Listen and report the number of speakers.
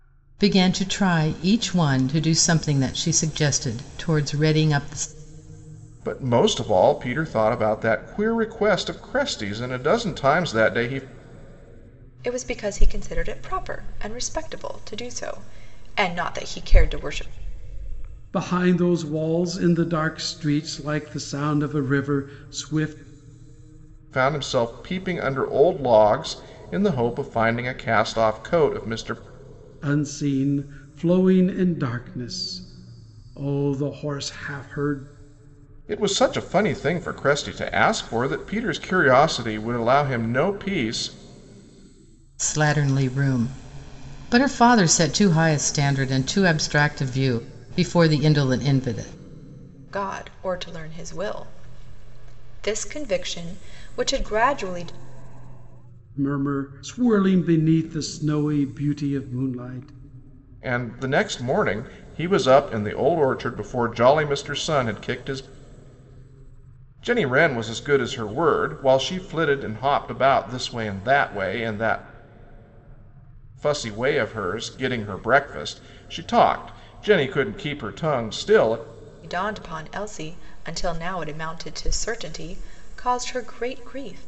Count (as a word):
four